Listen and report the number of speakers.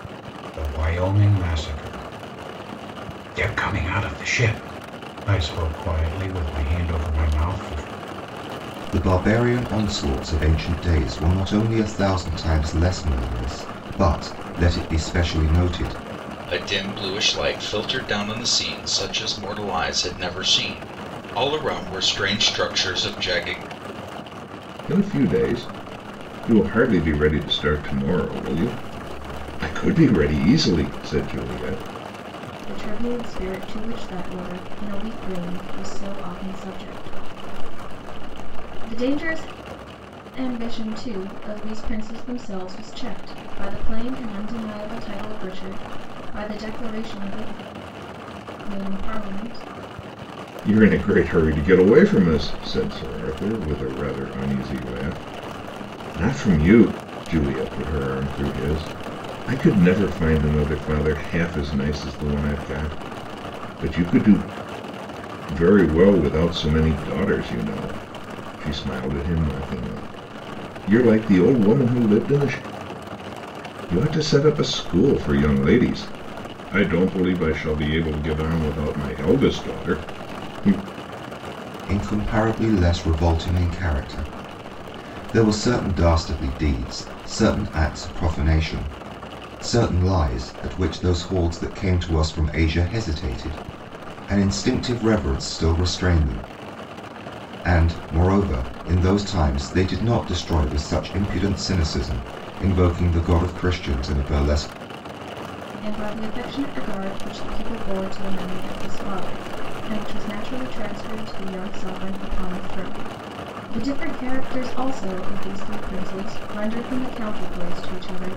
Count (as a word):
five